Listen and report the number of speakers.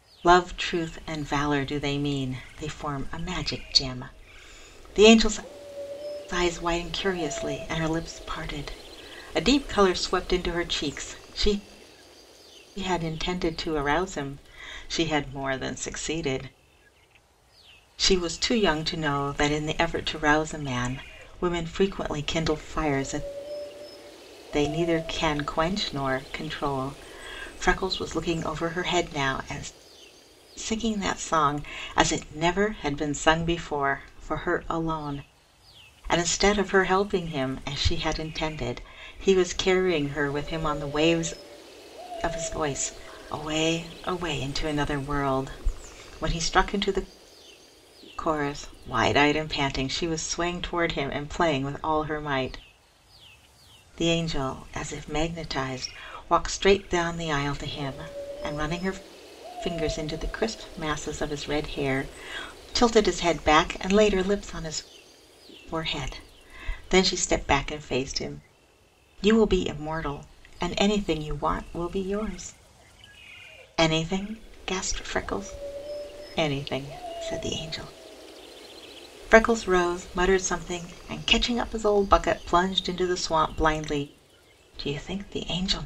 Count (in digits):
1